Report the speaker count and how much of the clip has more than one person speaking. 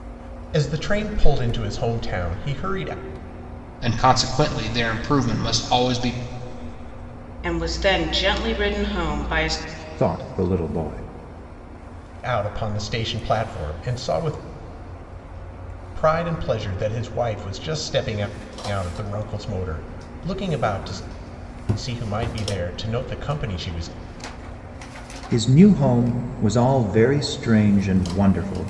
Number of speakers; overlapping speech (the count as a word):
four, no overlap